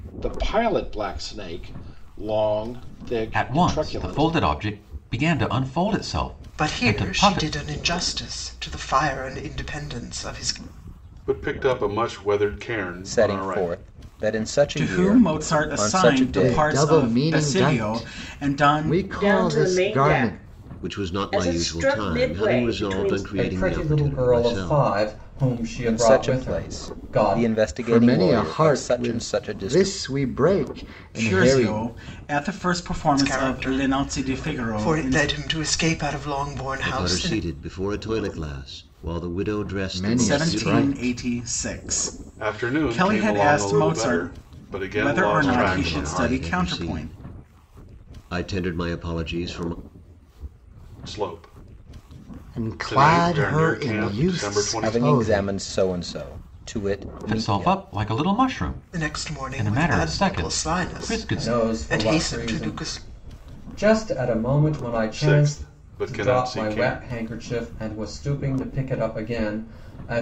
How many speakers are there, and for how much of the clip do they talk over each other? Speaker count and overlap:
ten, about 49%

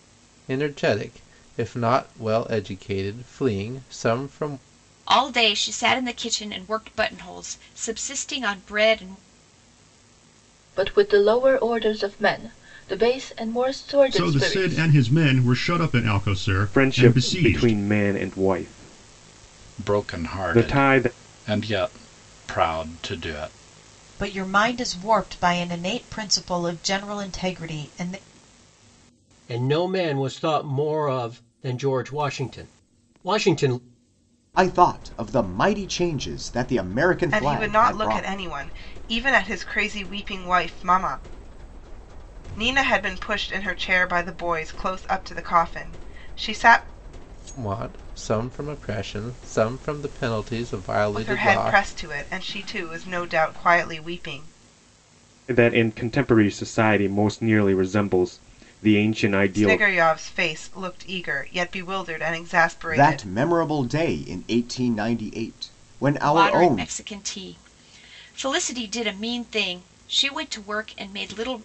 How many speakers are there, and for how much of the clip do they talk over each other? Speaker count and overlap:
ten, about 9%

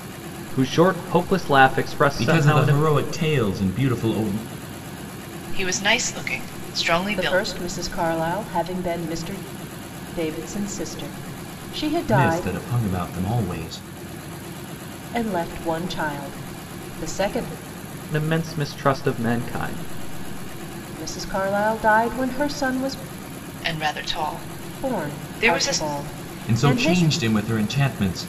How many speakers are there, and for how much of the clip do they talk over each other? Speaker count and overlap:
four, about 12%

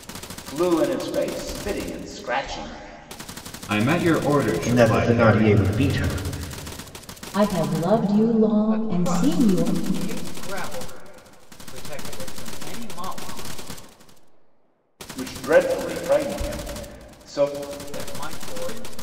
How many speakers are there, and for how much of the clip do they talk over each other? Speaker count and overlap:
five, about 10%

